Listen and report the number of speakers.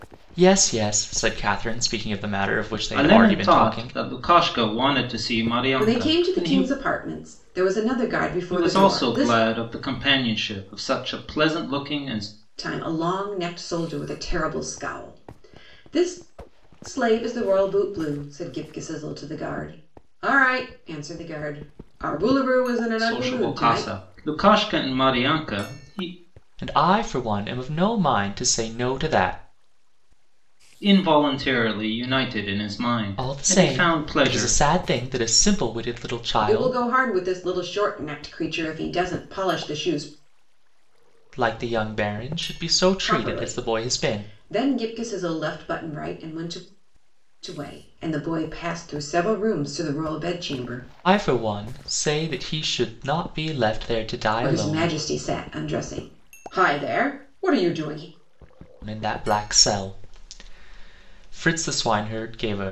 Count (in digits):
3